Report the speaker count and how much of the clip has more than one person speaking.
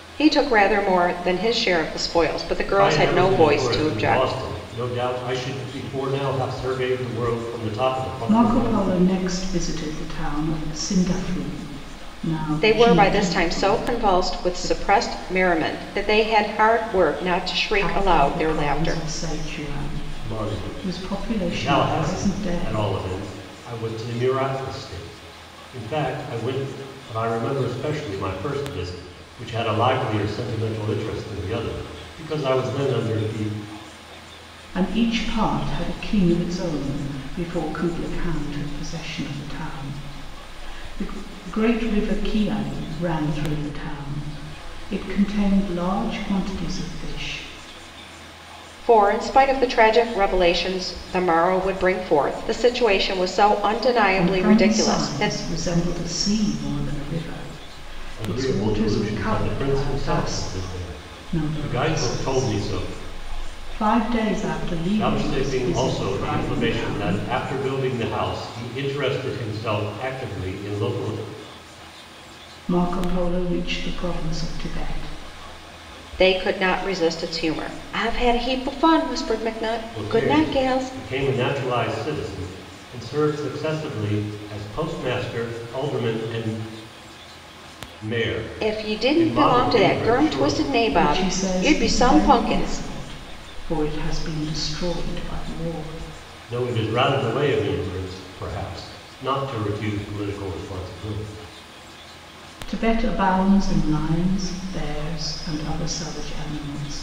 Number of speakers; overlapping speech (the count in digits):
3, about 20%